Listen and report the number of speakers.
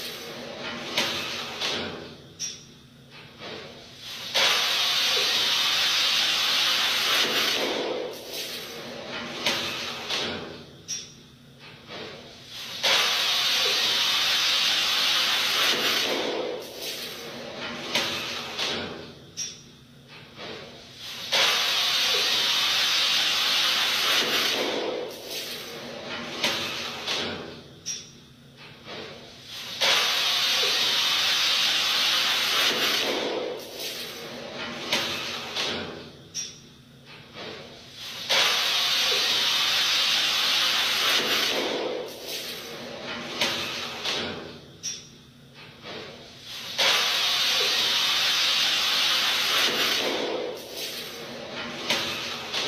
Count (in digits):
0